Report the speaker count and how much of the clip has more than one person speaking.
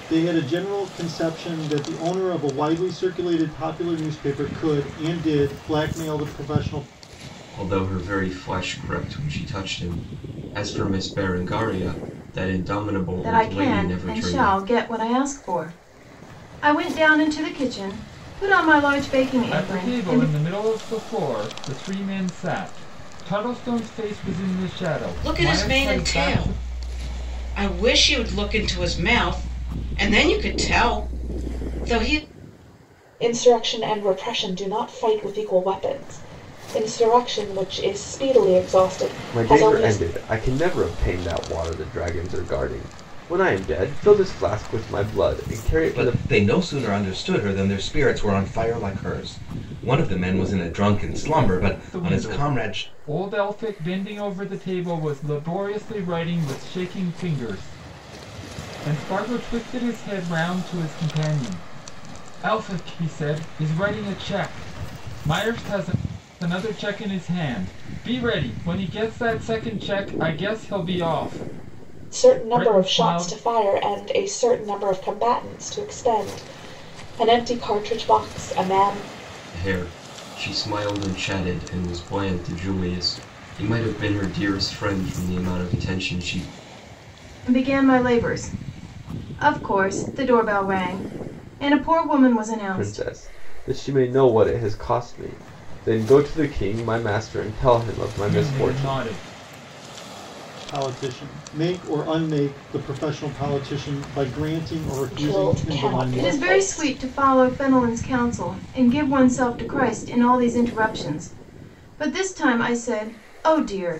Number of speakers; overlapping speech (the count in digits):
8, about 9%